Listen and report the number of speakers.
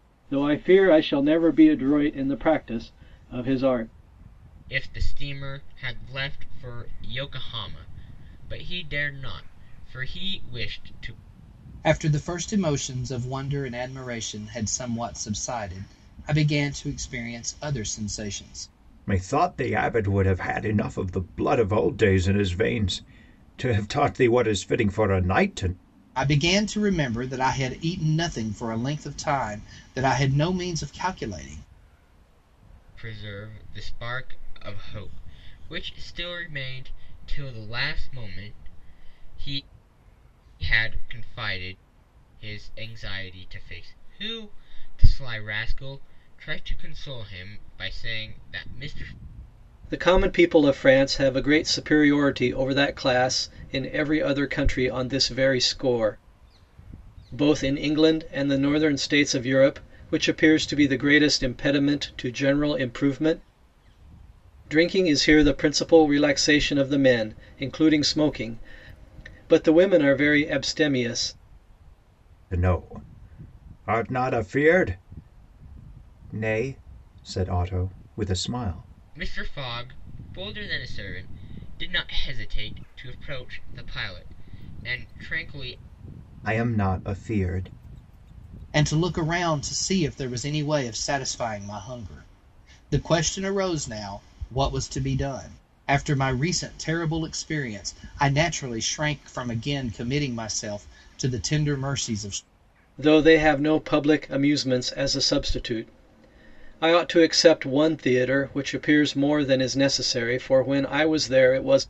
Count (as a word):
four